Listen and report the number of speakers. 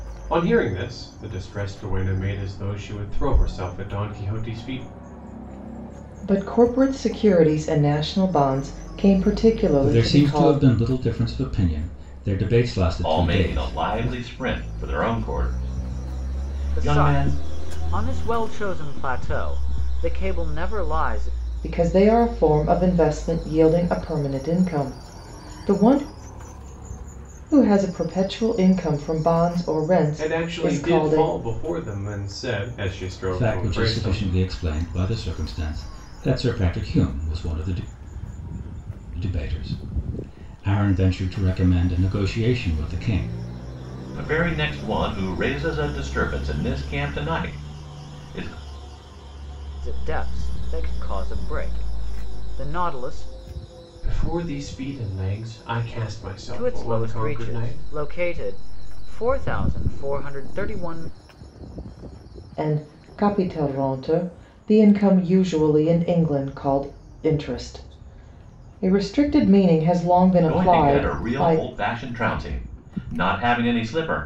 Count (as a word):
five